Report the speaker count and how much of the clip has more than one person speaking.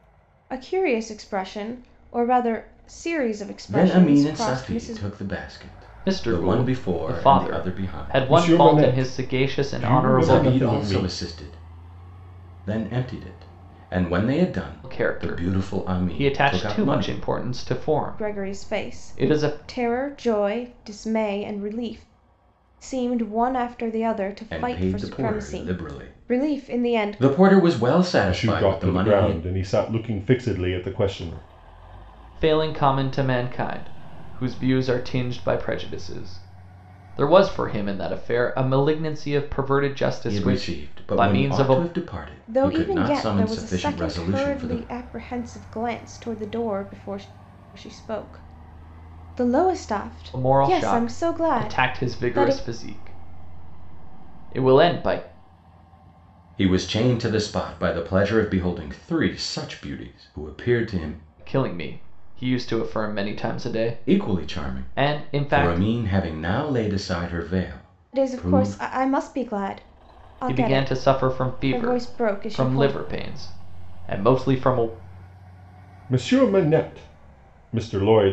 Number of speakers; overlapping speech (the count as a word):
four, about 33%